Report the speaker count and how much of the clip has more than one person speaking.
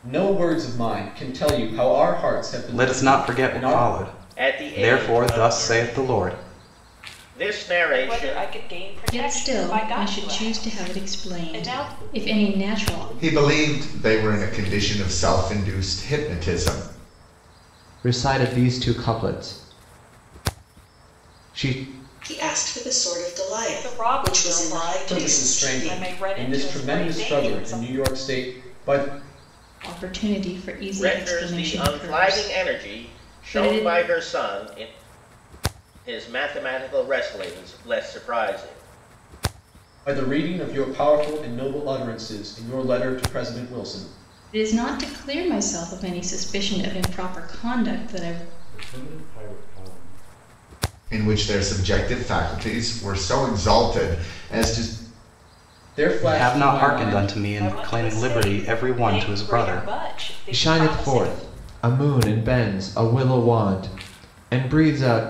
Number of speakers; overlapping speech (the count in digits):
9, about 36%